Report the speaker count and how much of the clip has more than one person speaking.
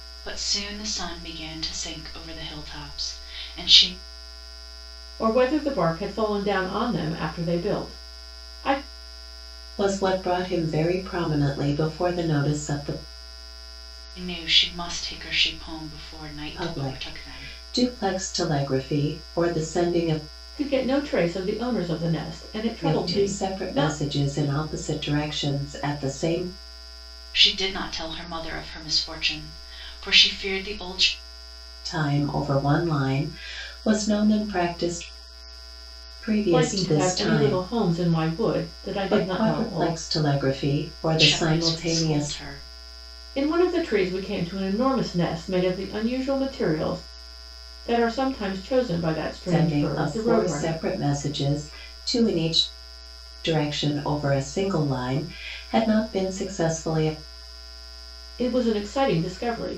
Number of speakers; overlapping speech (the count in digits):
3, about 12%